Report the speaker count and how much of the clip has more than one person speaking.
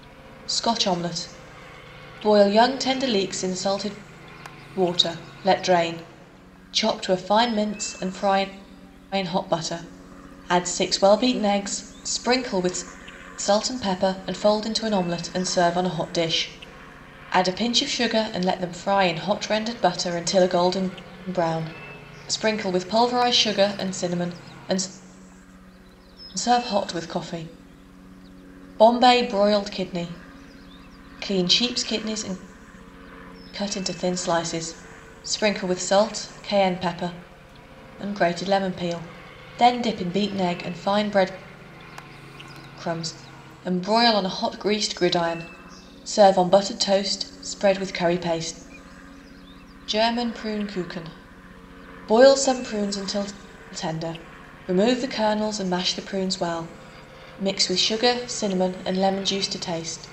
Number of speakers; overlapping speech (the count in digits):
1, no overlap